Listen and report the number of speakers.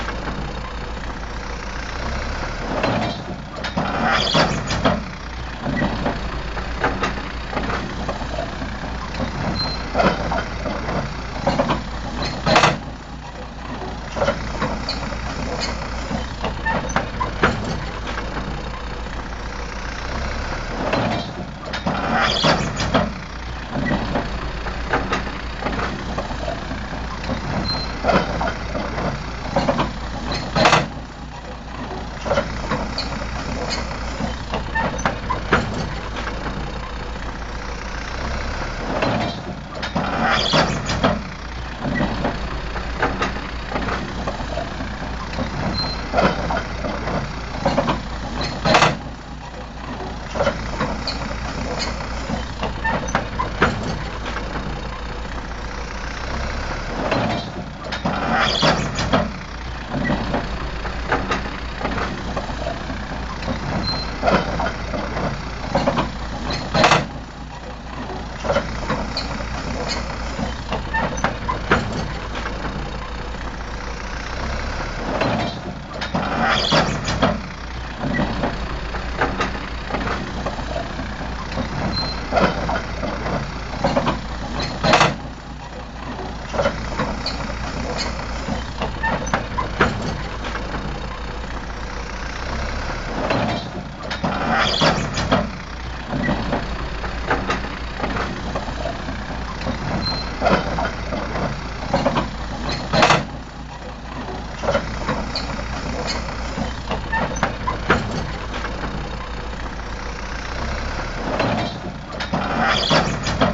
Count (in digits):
0